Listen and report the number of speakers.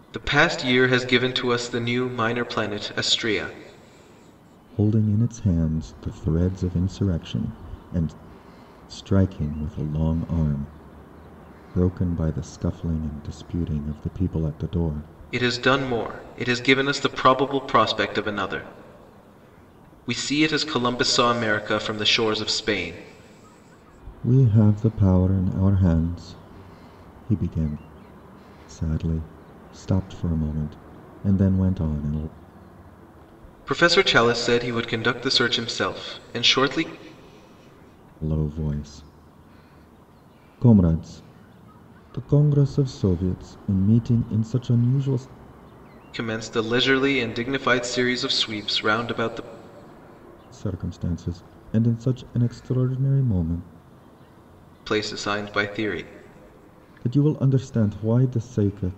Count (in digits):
2